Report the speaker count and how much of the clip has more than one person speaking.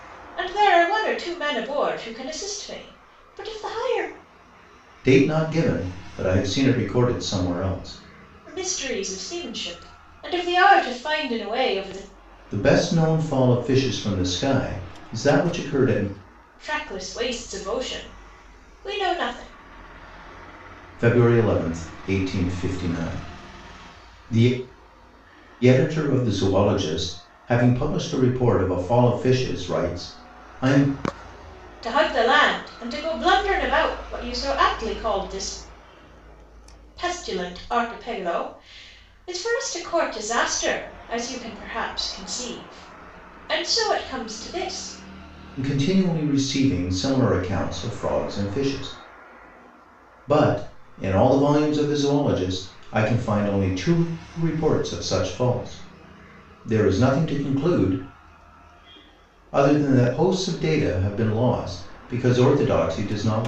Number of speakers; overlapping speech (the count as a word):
two, no overlap